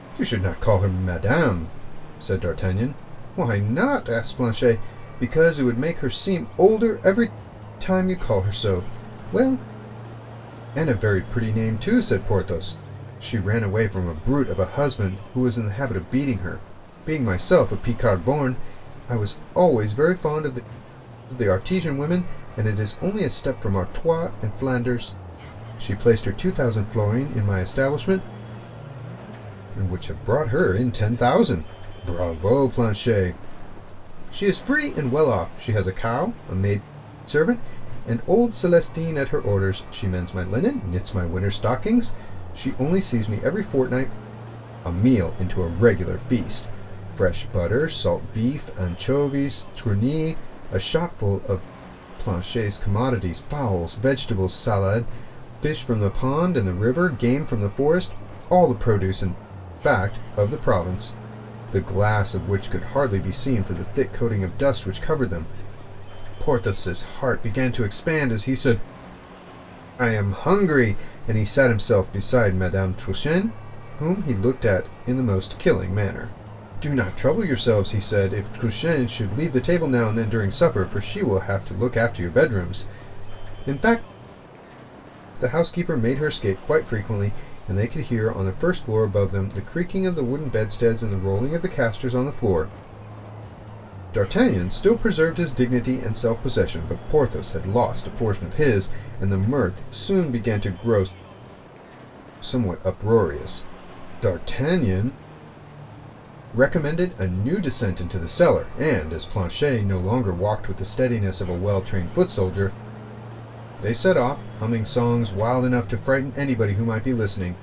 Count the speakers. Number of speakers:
one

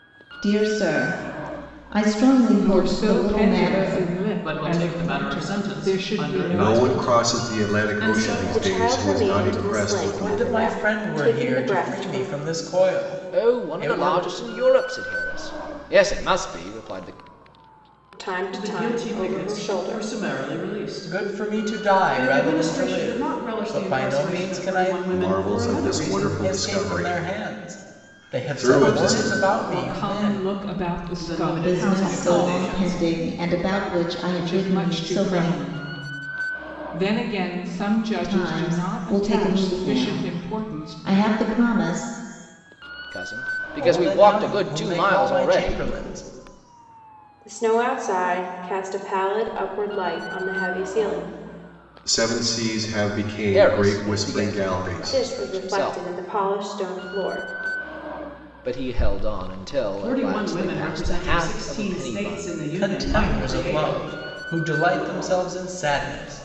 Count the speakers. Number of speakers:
seven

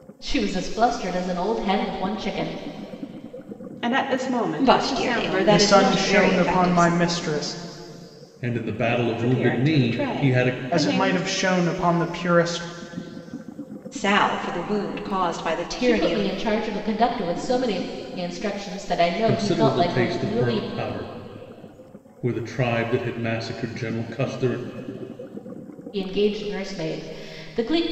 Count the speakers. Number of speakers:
five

